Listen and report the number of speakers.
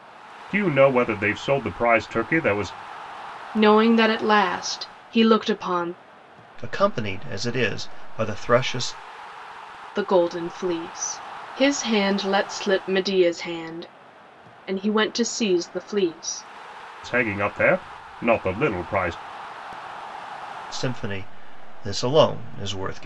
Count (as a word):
three